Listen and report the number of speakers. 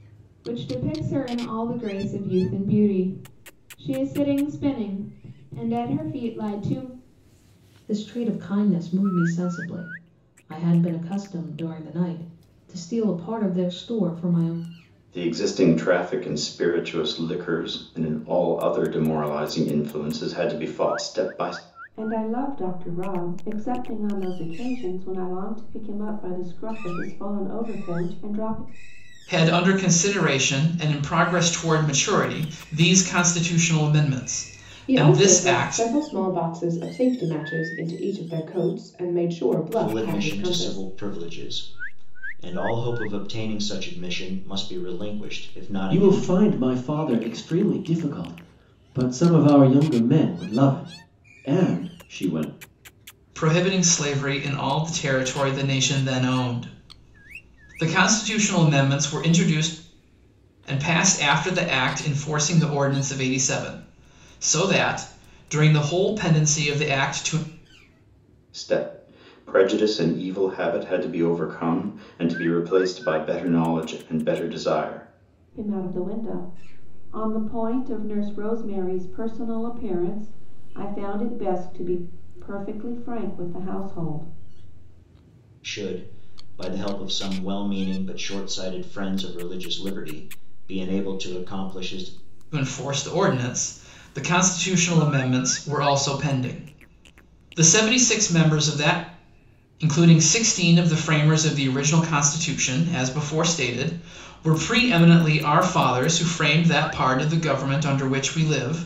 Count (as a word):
eight